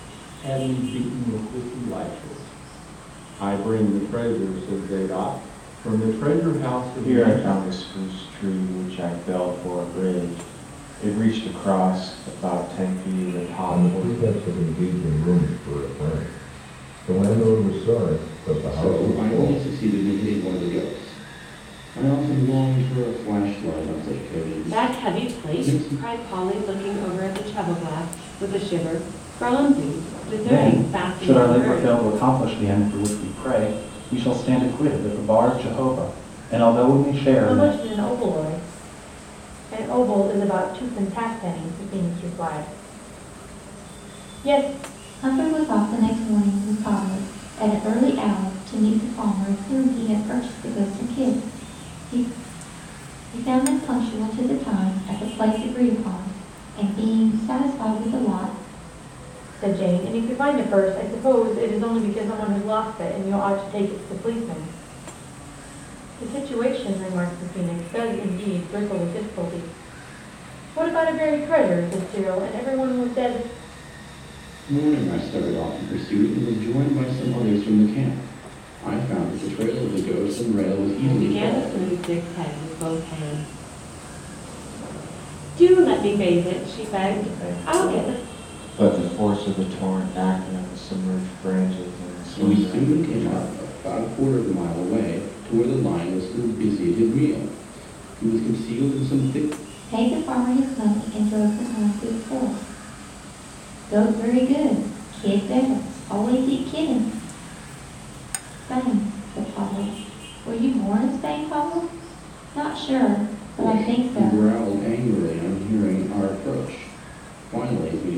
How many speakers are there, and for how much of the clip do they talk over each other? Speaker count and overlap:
eight, about 8%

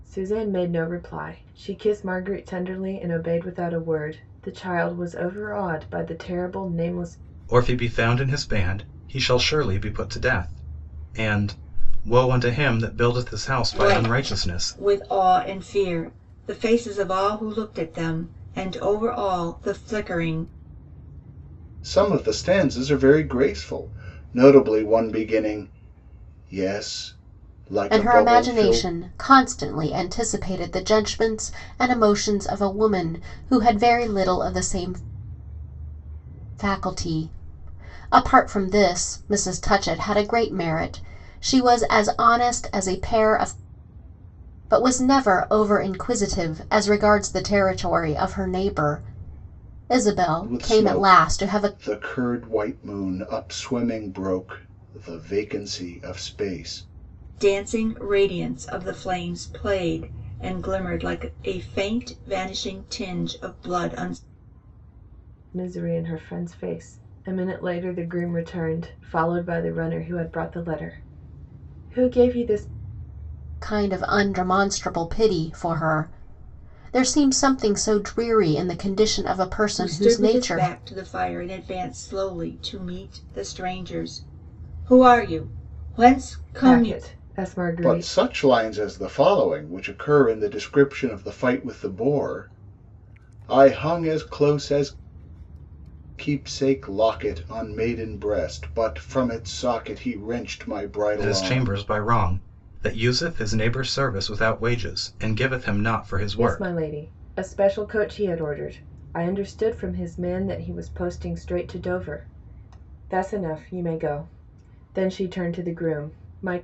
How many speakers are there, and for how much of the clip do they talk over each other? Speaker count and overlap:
five, about 6%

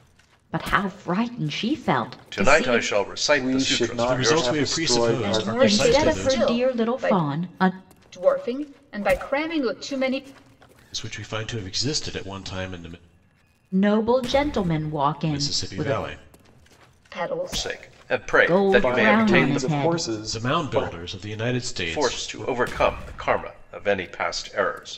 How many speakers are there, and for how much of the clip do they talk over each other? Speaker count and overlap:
five, about 36%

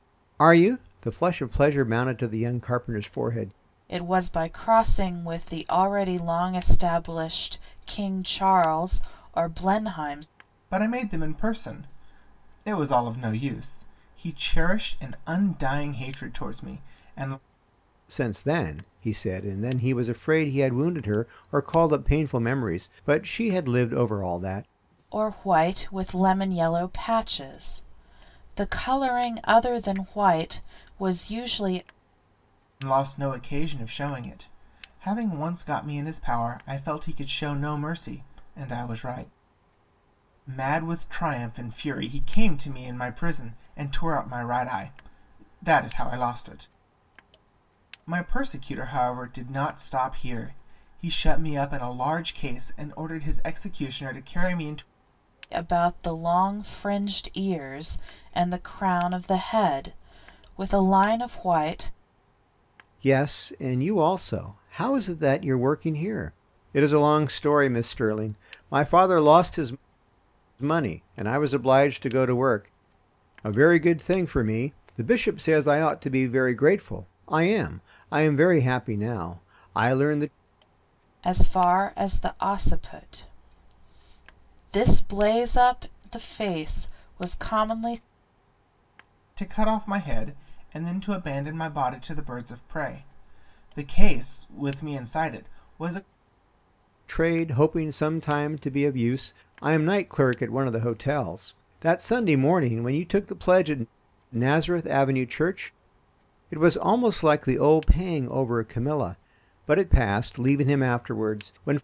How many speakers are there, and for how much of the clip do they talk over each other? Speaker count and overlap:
three, no overlap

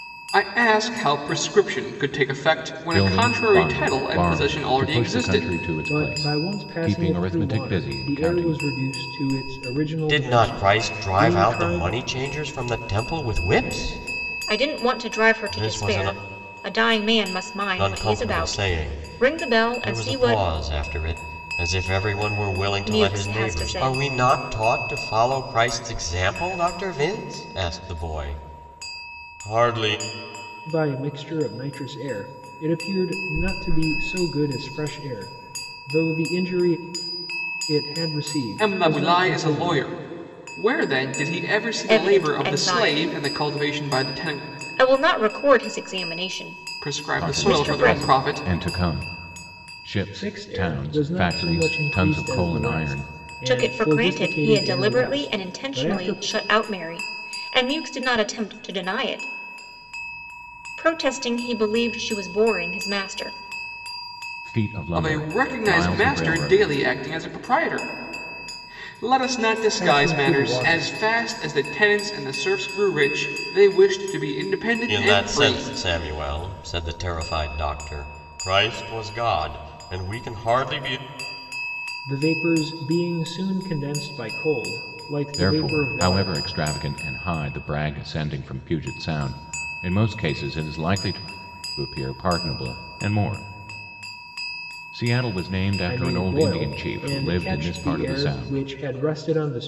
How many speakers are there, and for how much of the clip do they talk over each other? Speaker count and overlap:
five, about 32%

